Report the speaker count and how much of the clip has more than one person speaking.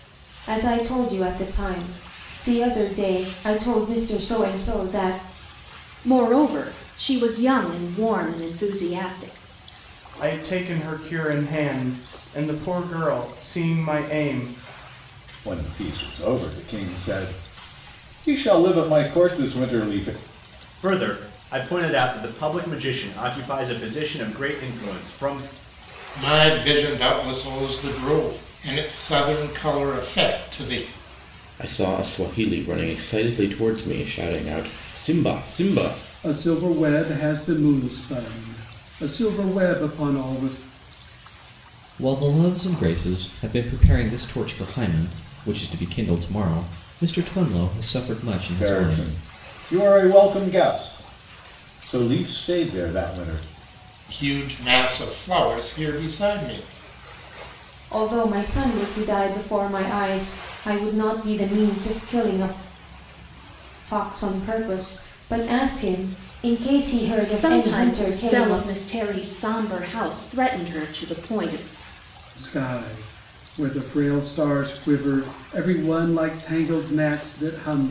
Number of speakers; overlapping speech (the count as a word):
nine, about 2%